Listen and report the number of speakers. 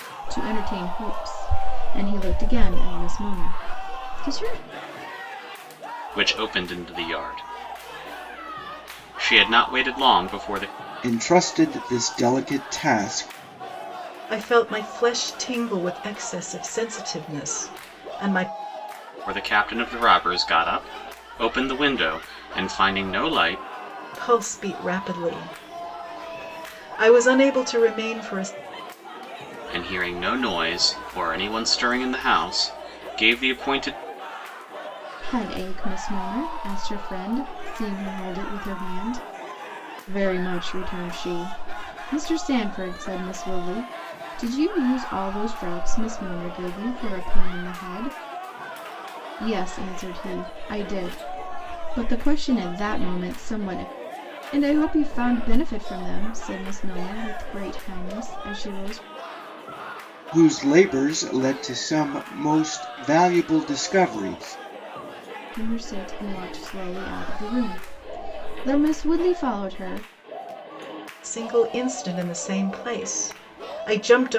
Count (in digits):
4